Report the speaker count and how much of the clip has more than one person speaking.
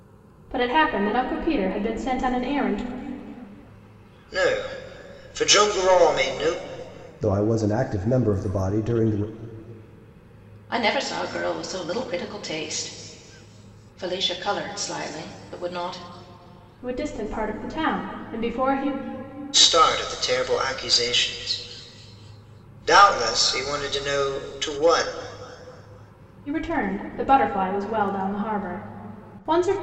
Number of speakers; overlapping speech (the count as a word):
four, no overlap